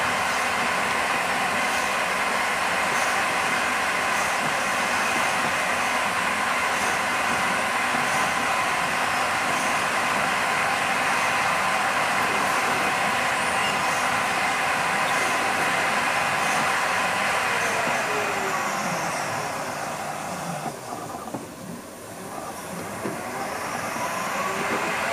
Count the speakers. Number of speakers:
zero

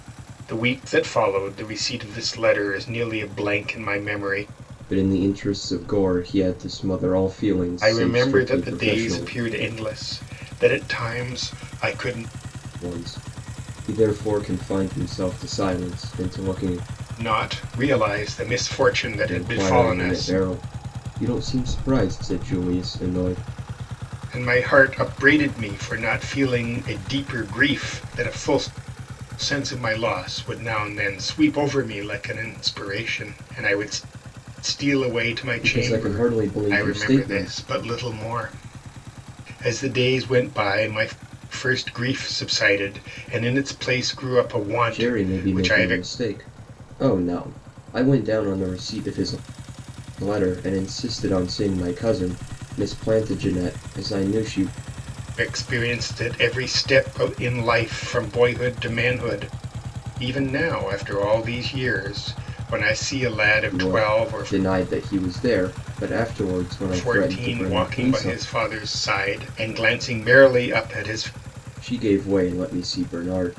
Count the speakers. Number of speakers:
two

